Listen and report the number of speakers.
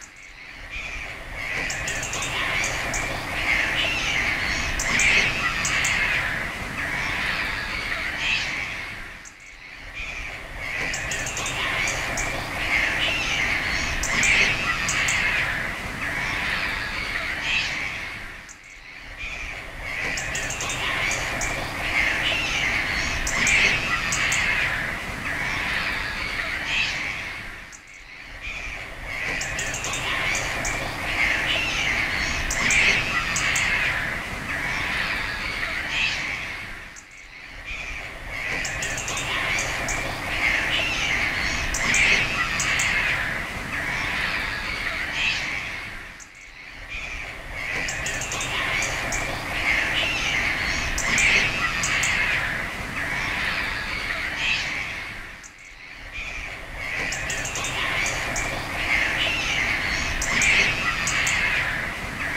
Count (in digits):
0